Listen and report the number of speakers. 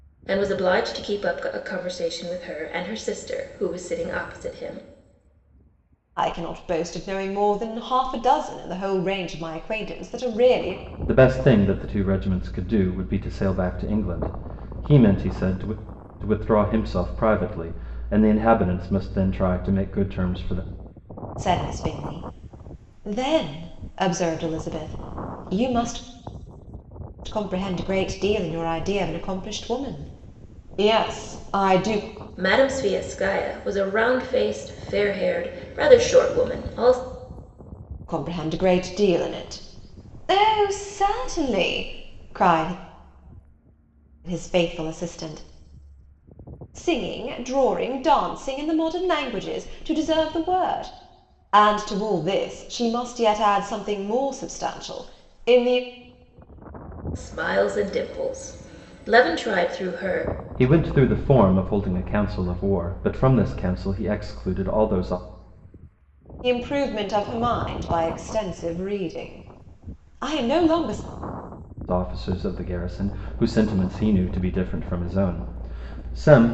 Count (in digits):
3